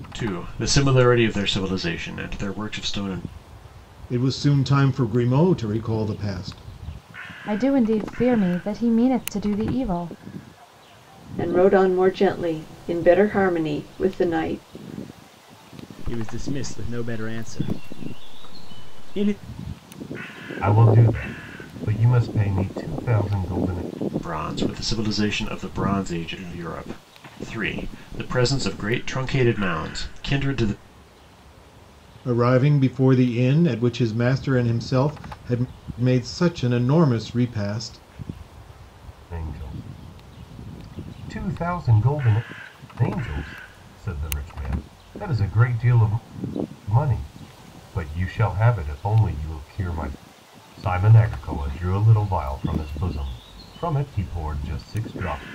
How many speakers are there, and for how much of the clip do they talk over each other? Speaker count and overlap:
6, no overlap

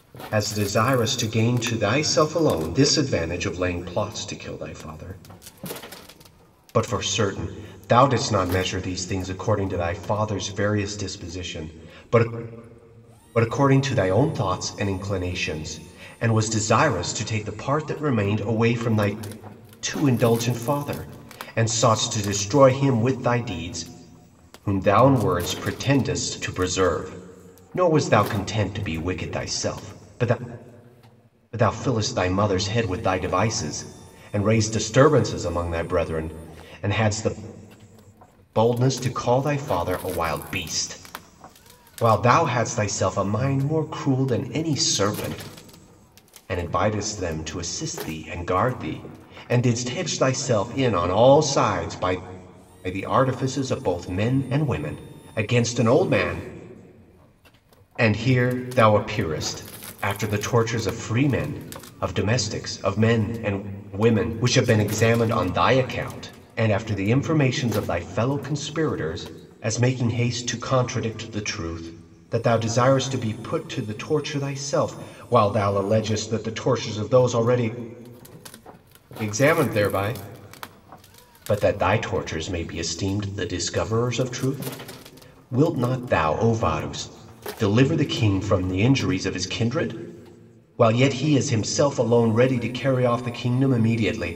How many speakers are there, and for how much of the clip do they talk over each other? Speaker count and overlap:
1, no overlap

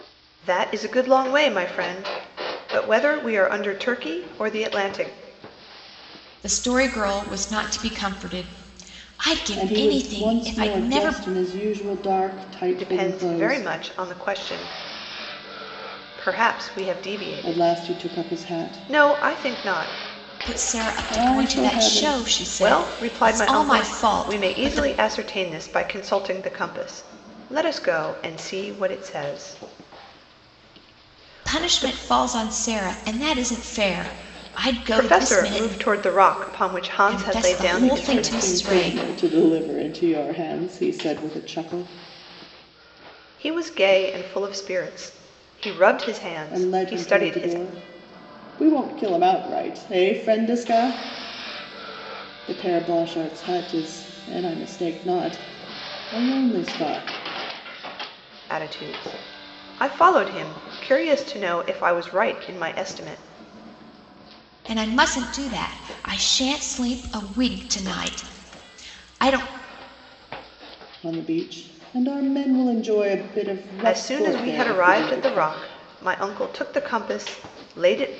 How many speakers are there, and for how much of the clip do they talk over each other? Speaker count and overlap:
3, about 21%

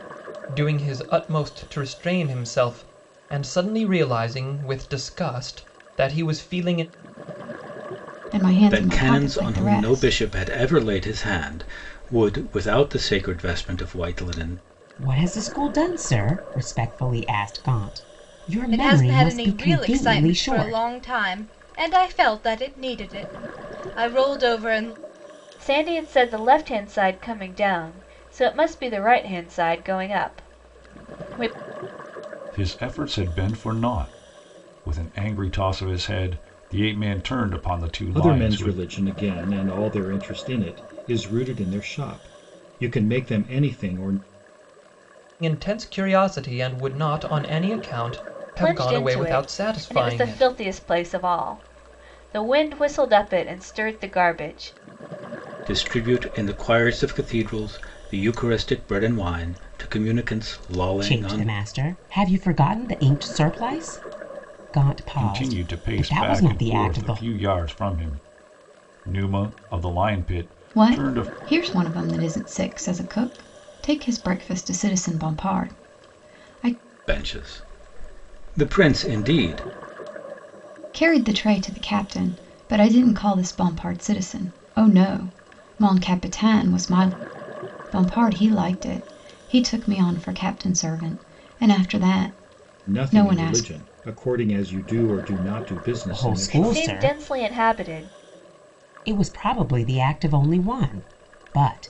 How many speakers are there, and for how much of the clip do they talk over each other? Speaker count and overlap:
8, about 11%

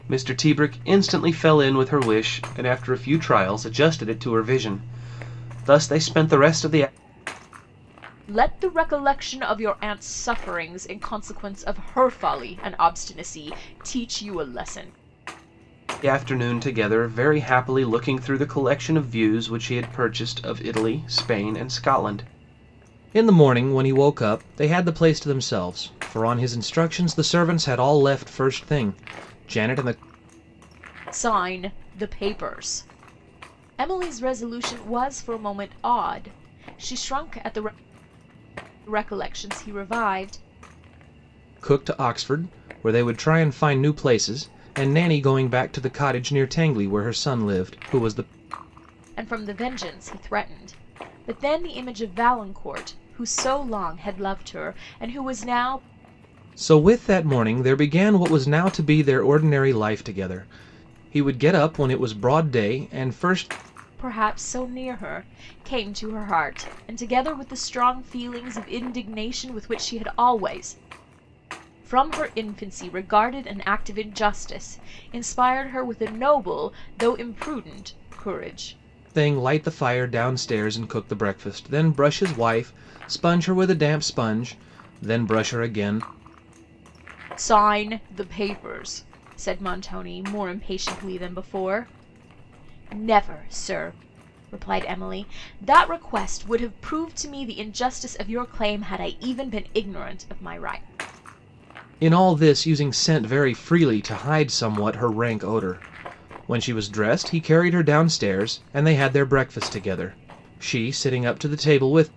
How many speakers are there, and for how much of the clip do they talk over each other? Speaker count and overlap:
2, no overlap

